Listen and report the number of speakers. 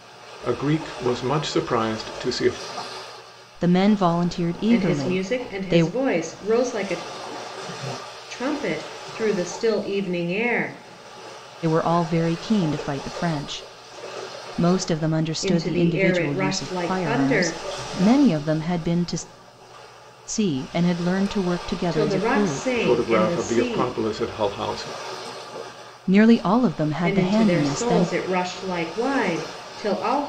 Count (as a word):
three